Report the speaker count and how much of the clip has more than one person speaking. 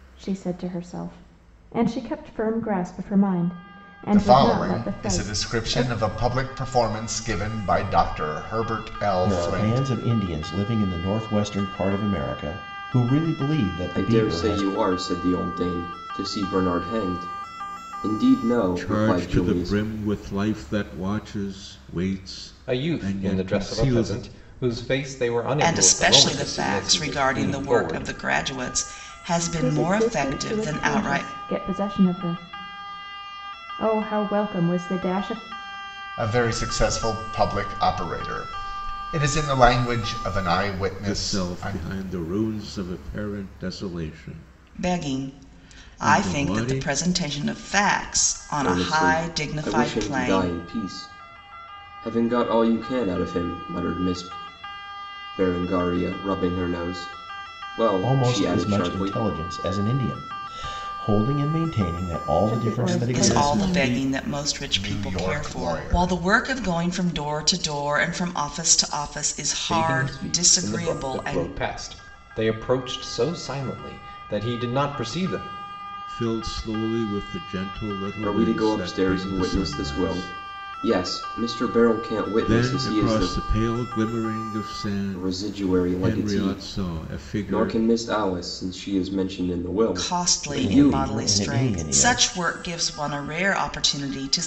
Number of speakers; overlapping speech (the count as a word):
seven, about 31%